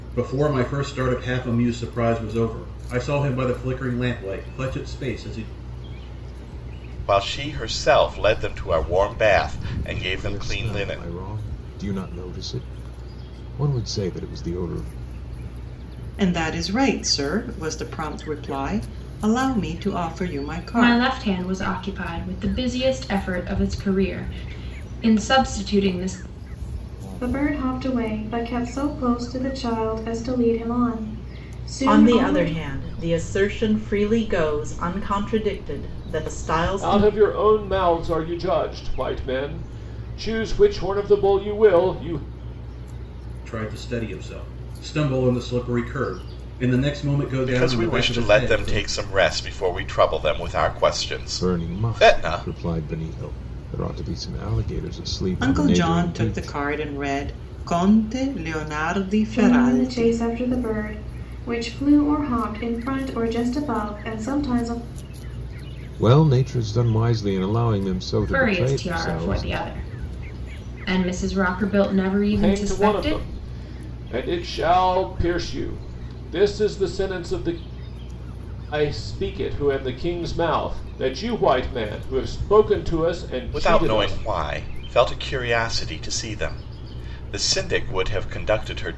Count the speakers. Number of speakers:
8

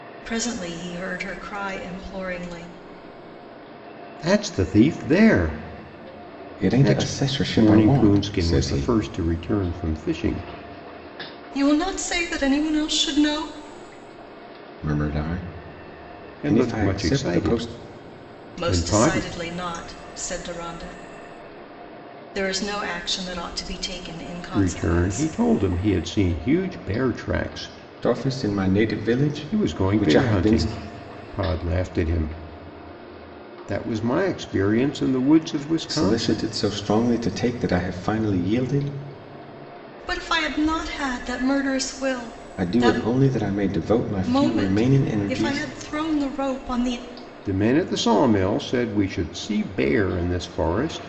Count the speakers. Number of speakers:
3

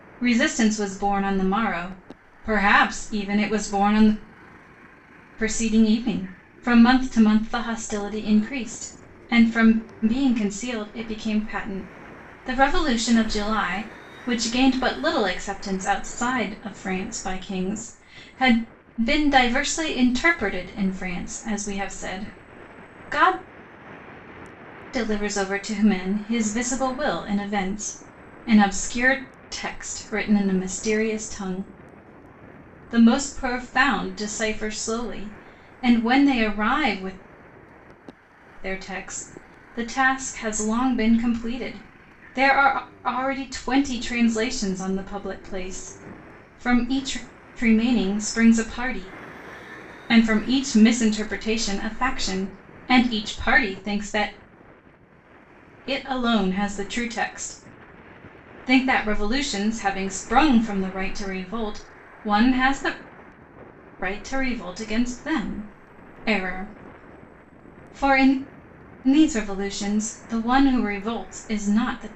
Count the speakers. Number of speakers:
1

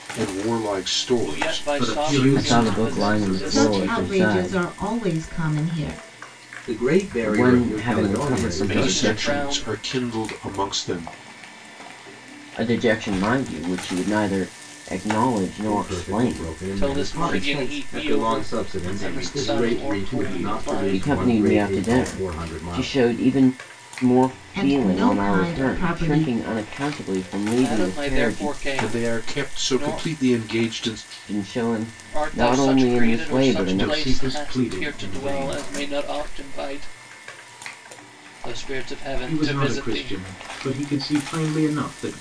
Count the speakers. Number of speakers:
6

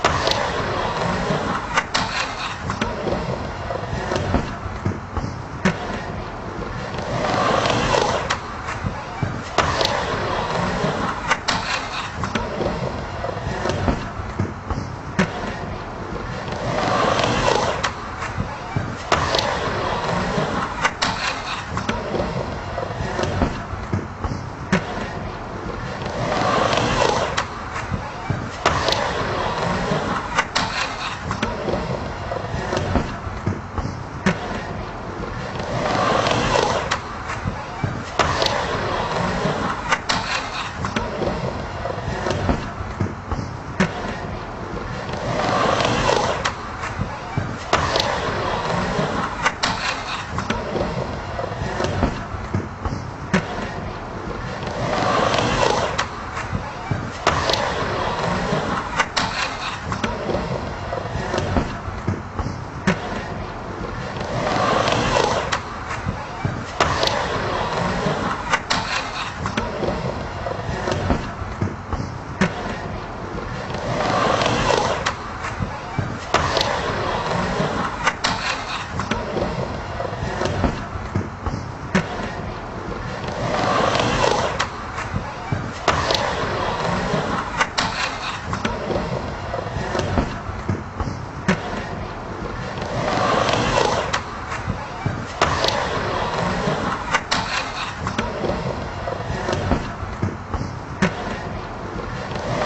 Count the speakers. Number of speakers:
0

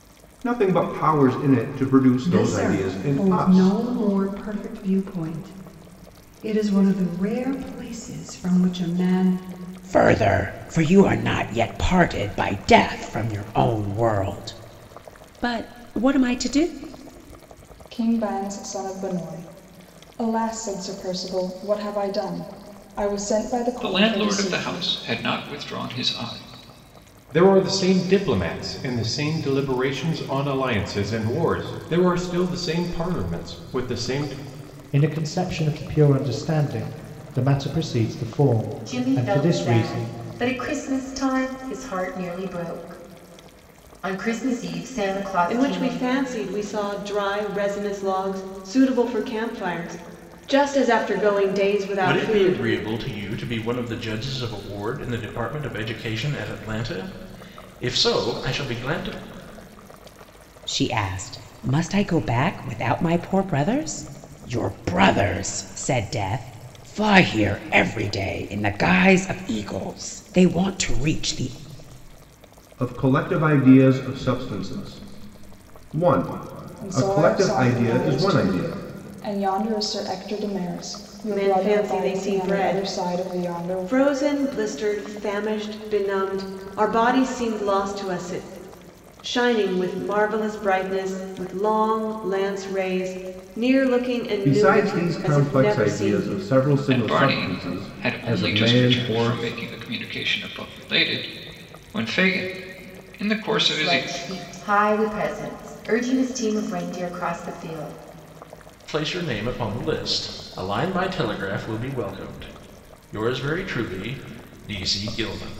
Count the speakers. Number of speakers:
10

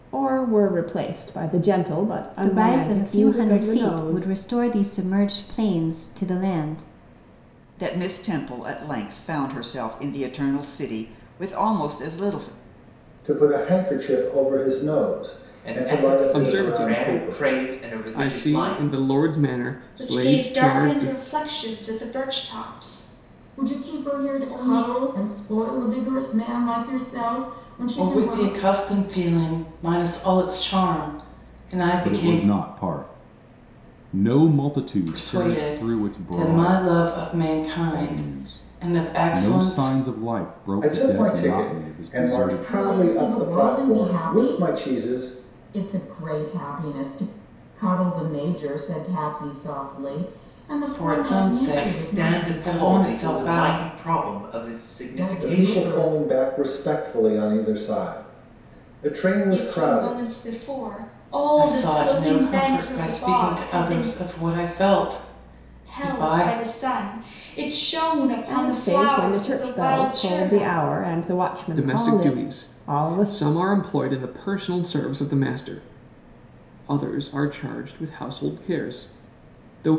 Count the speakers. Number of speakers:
10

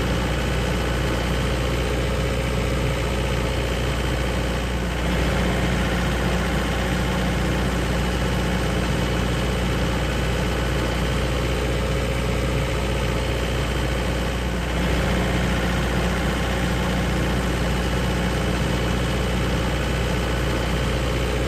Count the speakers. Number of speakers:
0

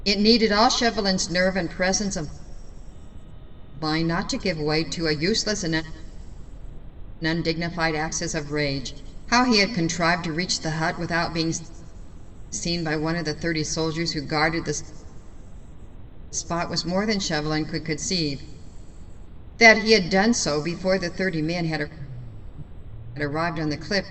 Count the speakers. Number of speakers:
1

